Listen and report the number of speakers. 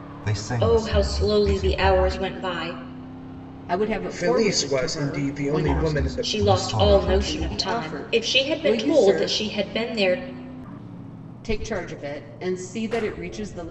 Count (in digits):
4